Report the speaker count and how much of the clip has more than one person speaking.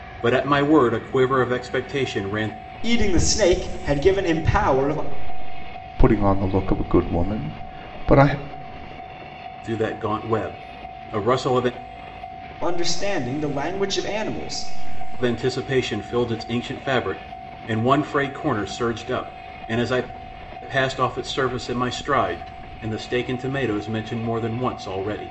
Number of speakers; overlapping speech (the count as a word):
three, no overlap